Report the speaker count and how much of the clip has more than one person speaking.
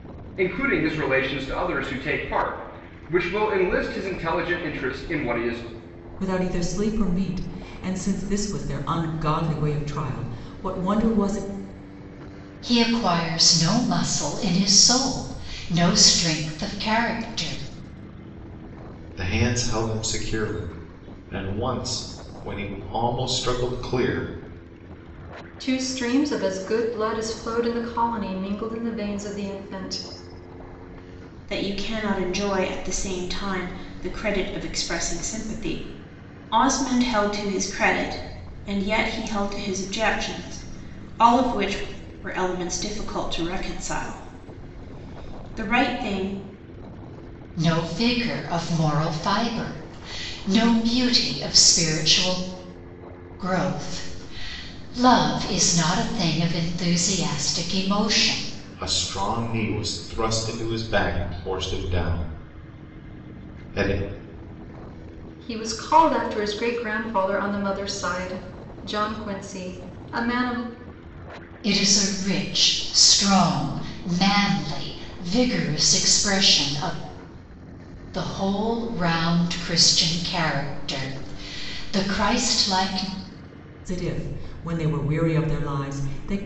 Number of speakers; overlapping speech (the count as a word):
six, no overlap